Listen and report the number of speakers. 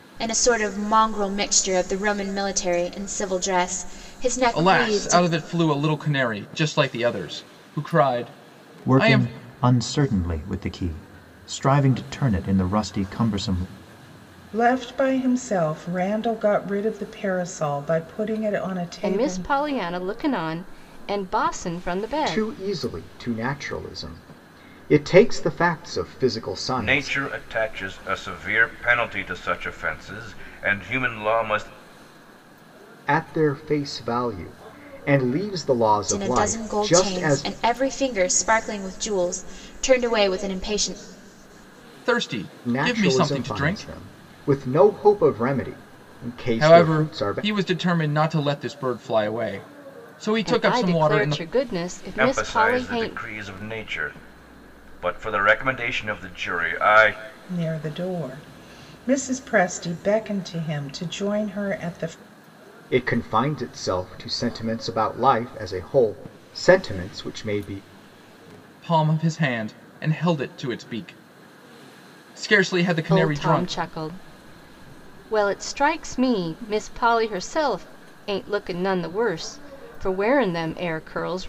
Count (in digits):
7